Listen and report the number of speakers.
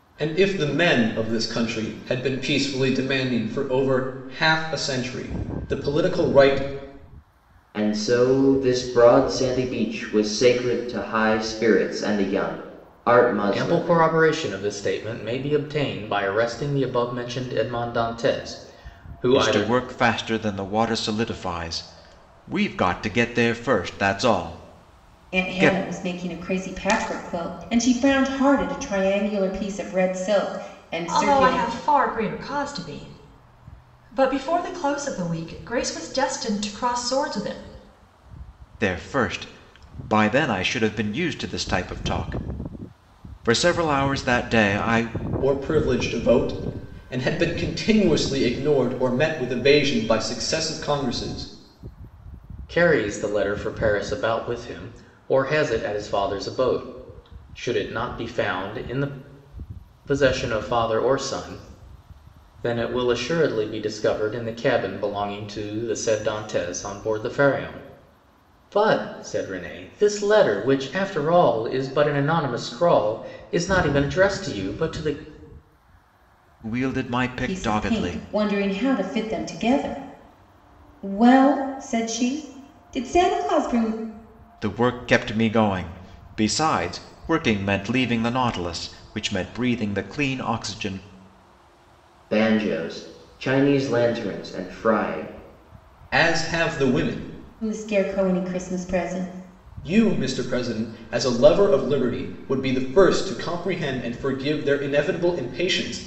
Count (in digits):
6